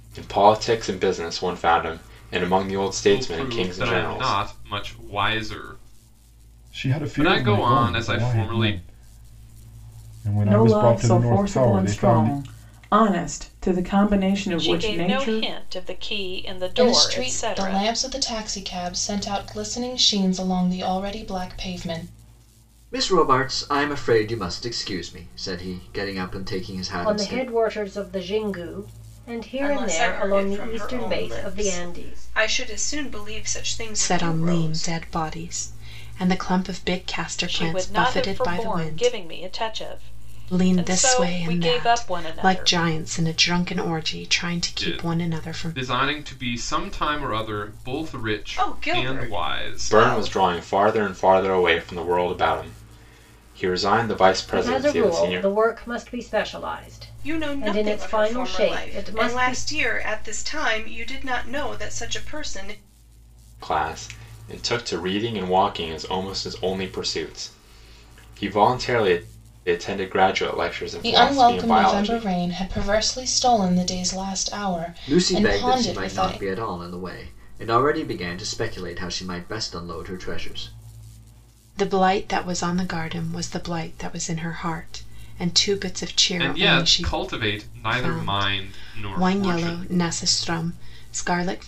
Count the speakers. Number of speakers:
10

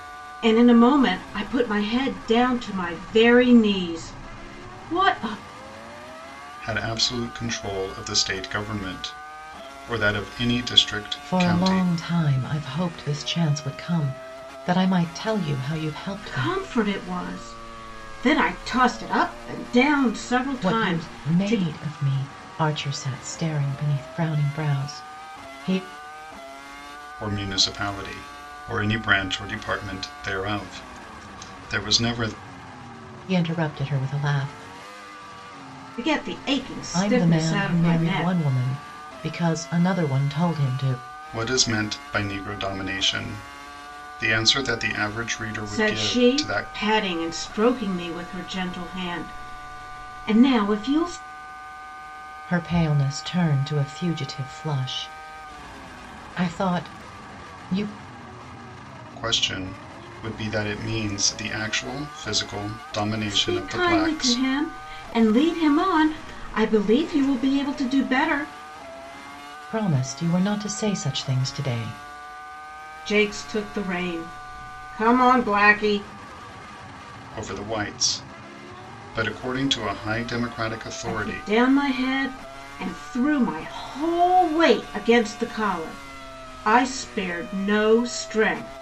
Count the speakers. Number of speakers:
3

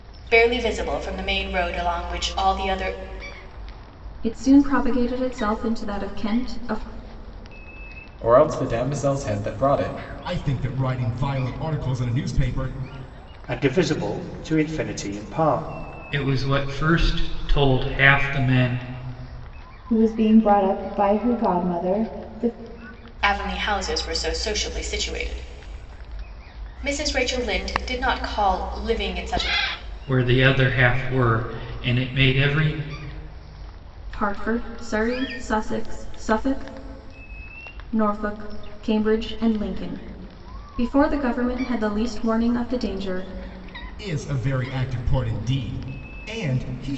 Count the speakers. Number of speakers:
7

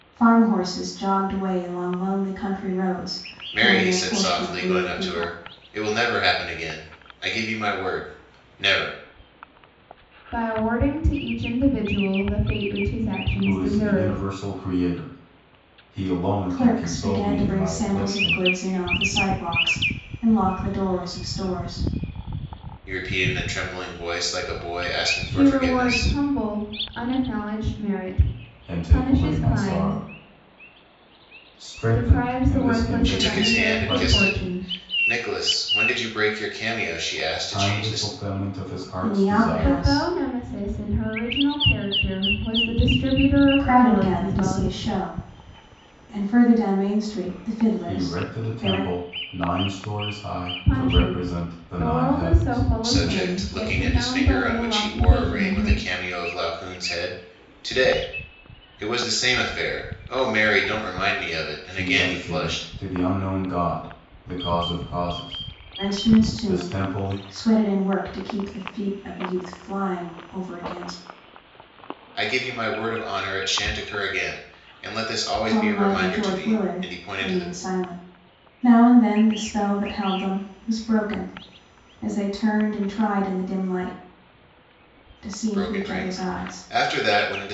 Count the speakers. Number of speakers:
4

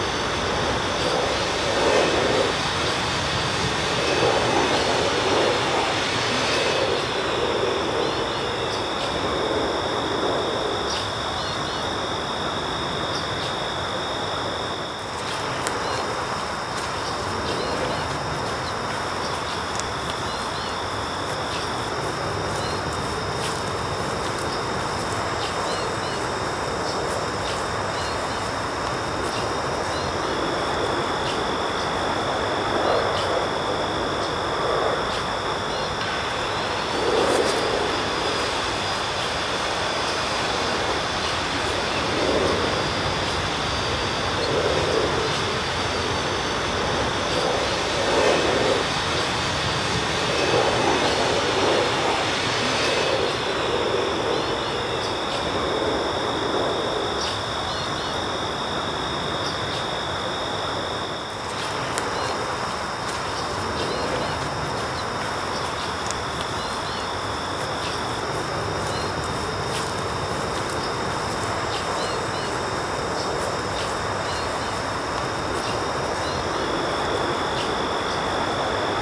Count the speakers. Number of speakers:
0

